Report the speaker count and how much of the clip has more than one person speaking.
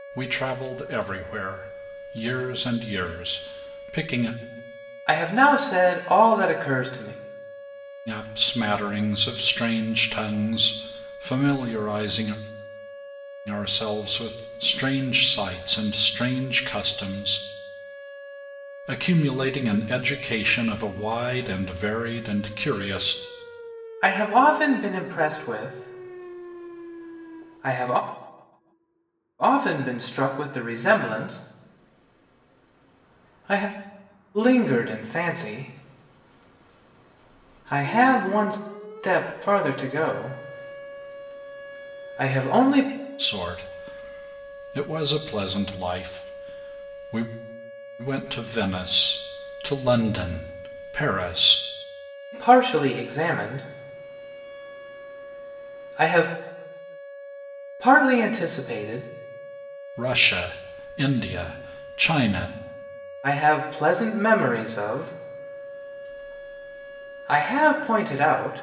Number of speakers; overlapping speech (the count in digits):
2, no overlap